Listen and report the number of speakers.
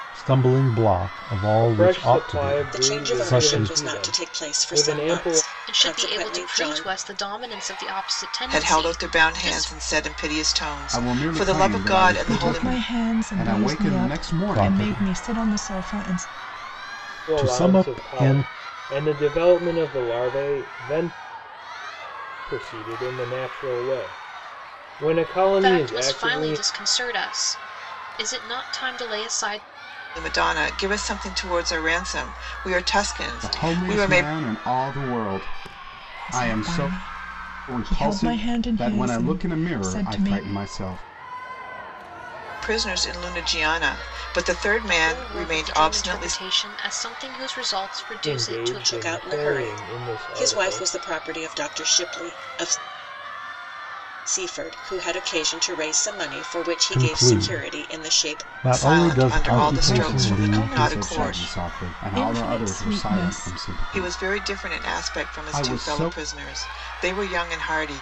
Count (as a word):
seven